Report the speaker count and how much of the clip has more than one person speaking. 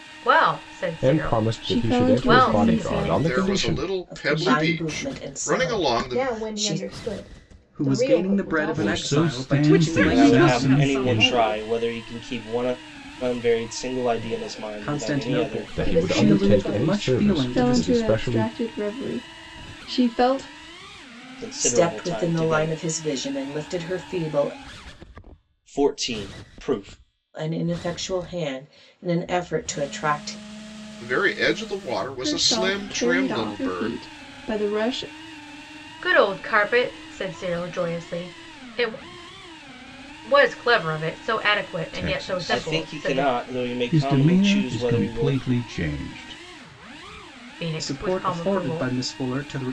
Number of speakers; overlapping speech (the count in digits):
10, about 44%